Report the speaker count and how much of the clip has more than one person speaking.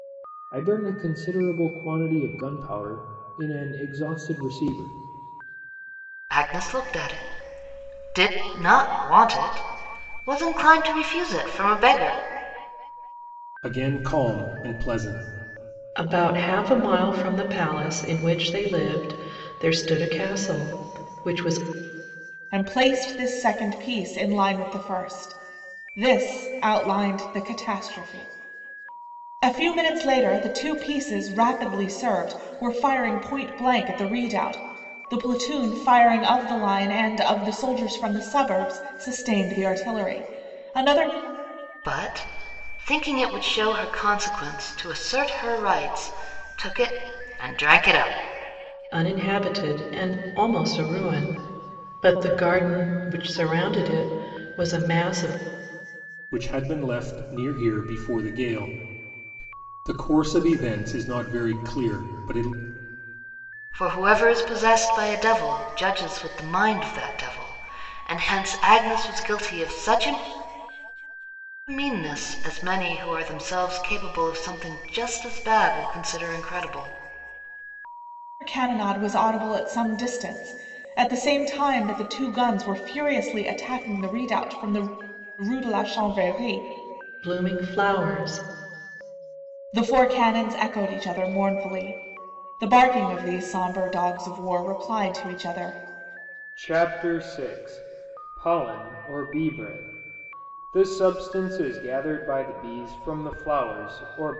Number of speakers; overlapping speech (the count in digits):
5, no overlap